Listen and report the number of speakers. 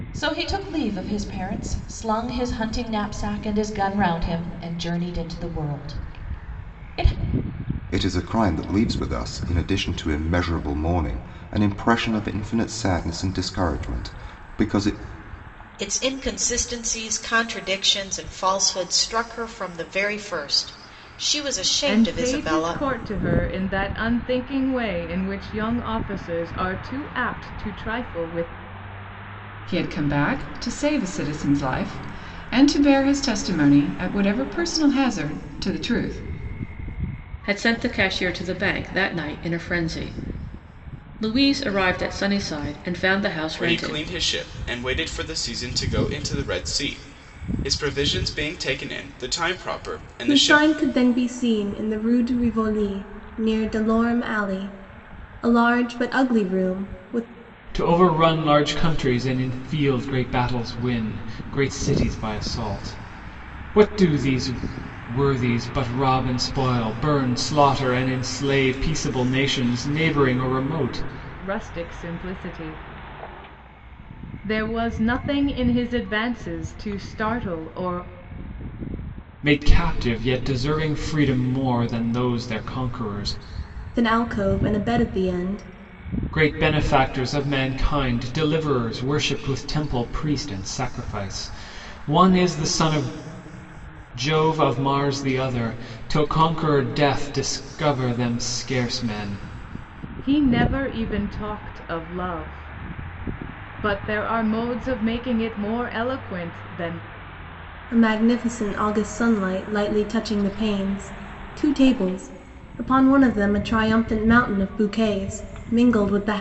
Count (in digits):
9